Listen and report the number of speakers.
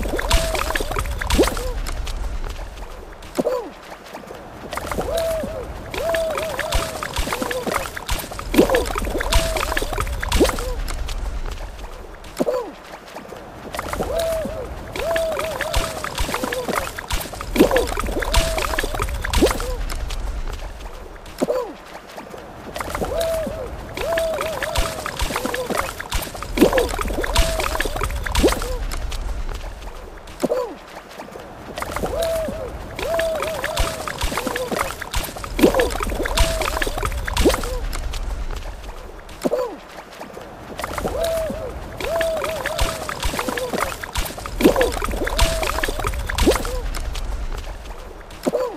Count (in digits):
0